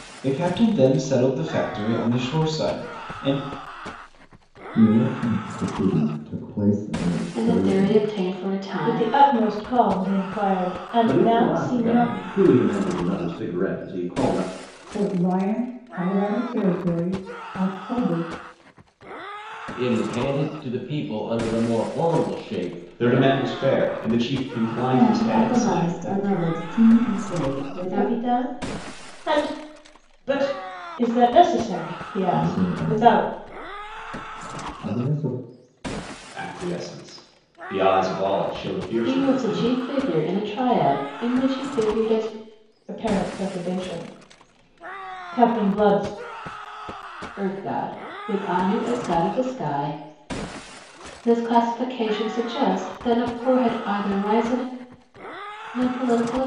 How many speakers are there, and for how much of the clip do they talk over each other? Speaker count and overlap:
9, about 10%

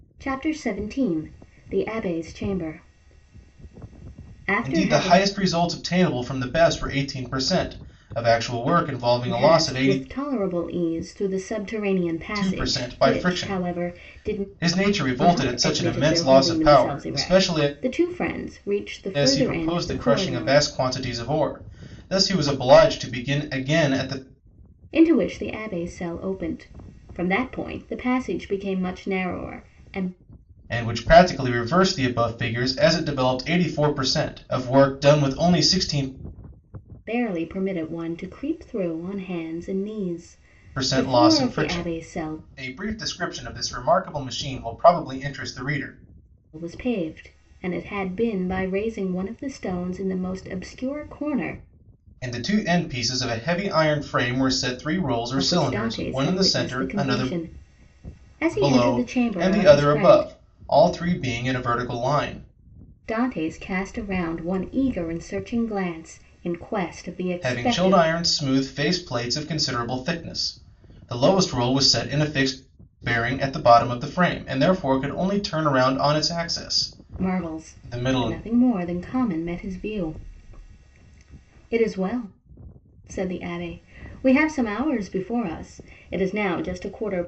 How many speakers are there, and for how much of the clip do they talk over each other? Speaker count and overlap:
2, about 17%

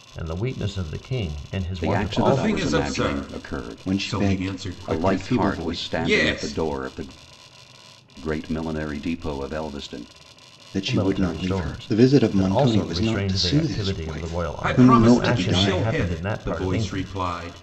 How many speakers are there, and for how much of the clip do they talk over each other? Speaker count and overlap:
4, about 63%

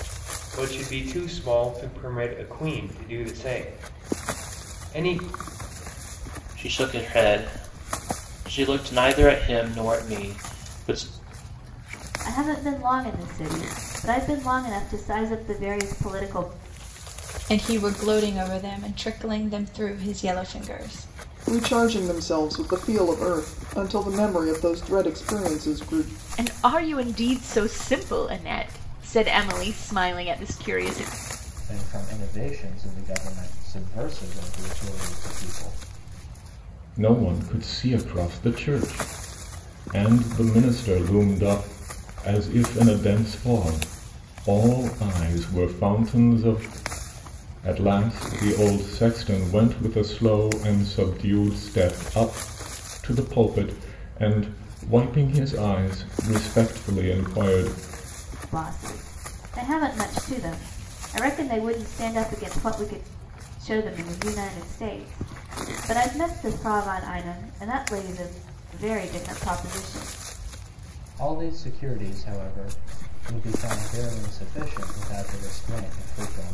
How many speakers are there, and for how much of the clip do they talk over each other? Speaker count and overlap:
8, no overlap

